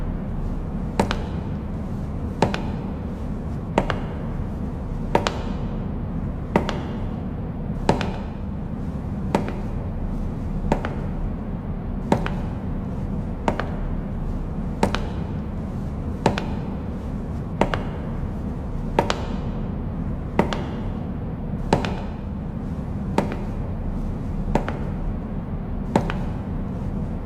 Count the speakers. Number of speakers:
zero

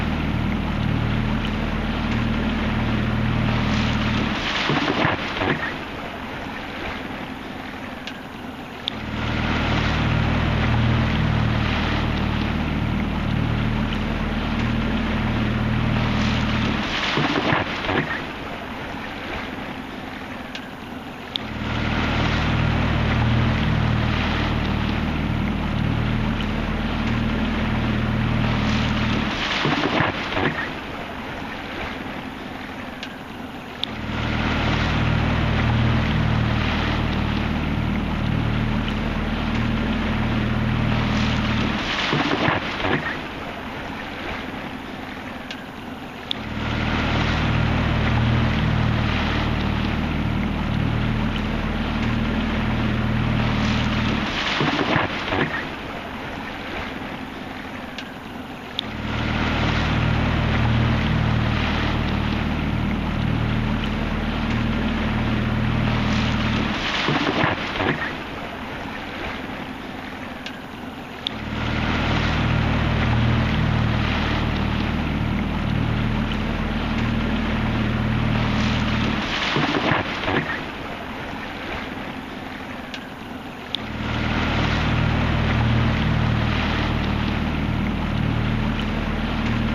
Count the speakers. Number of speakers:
zero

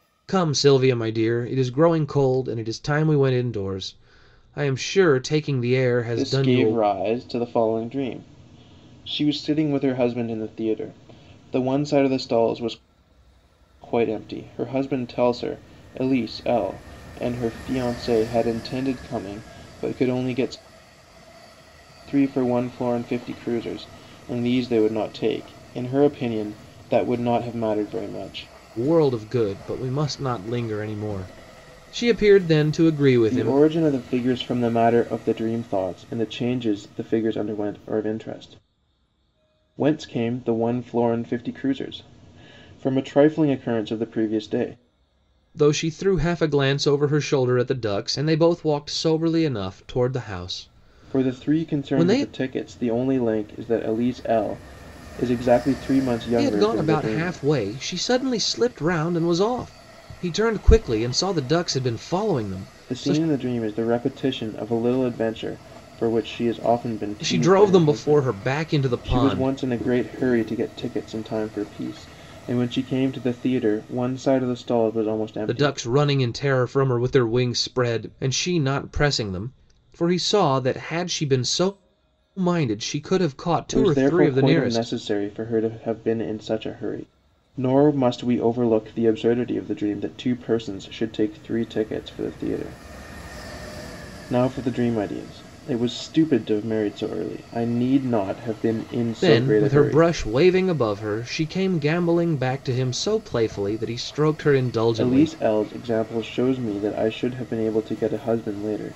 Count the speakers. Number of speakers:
two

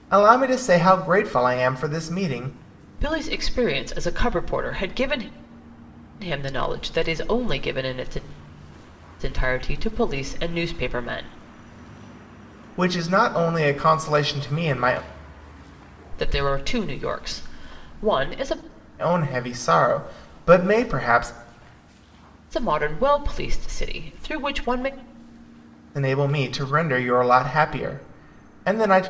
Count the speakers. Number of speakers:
two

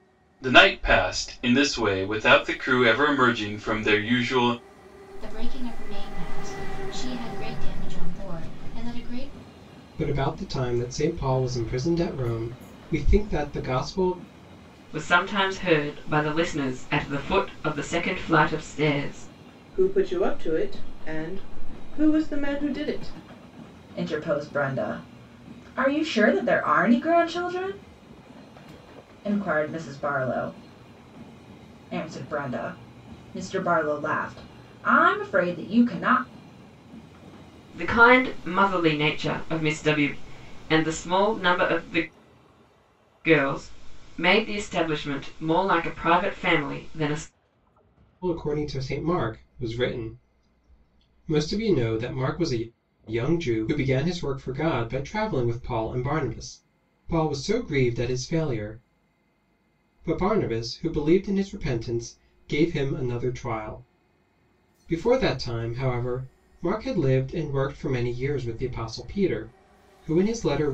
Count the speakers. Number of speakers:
six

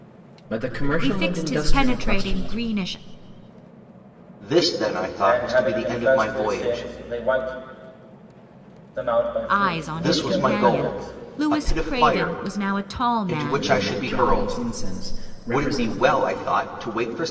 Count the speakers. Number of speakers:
four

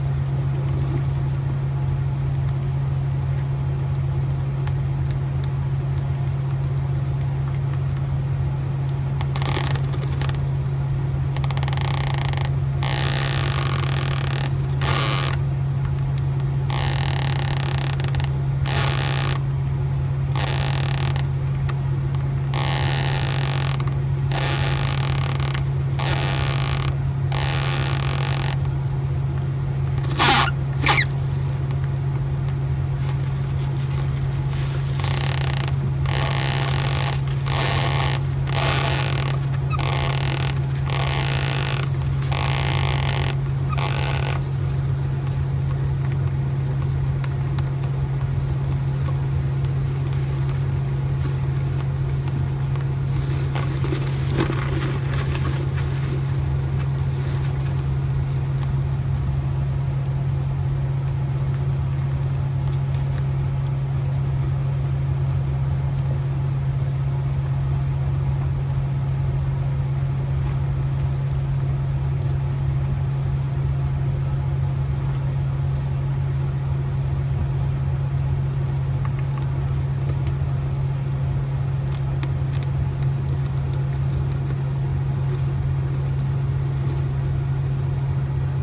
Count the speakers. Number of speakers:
zero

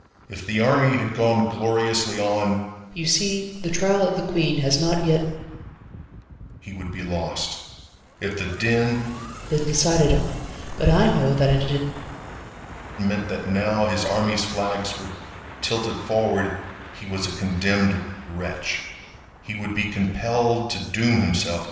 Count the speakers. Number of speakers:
two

